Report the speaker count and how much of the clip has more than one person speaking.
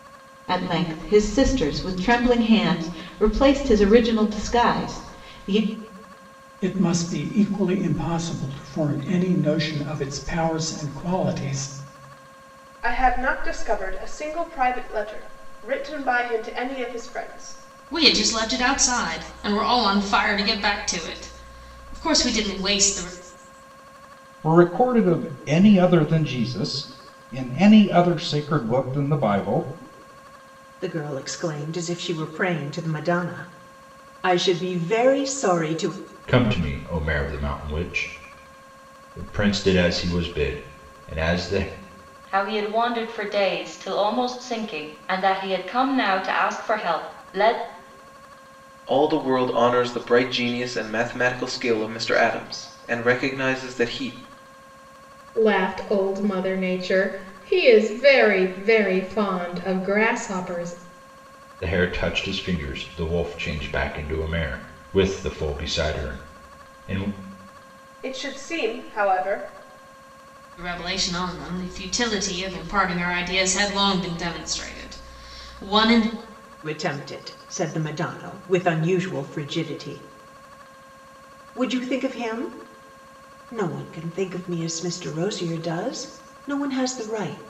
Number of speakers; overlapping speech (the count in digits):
10, no overlap